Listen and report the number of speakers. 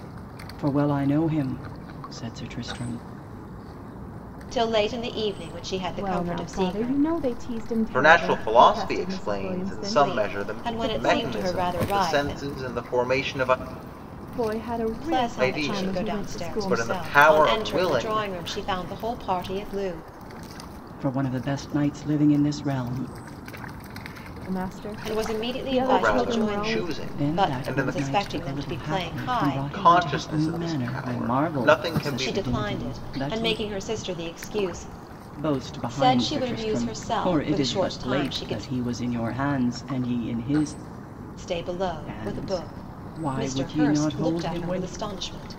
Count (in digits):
4